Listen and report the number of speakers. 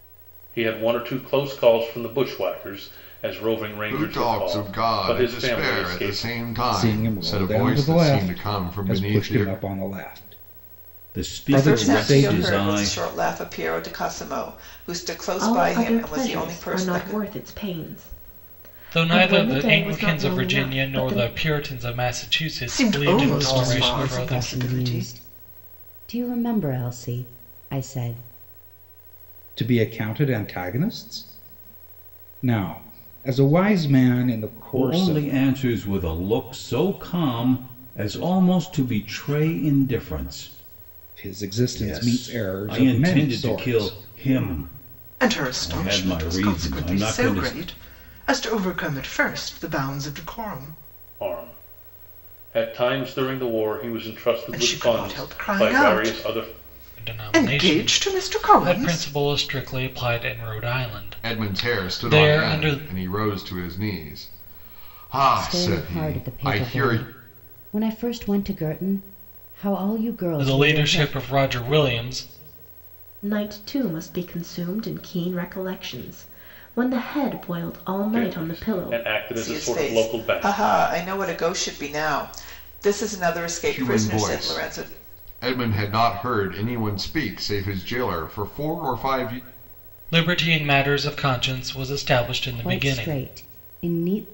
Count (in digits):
9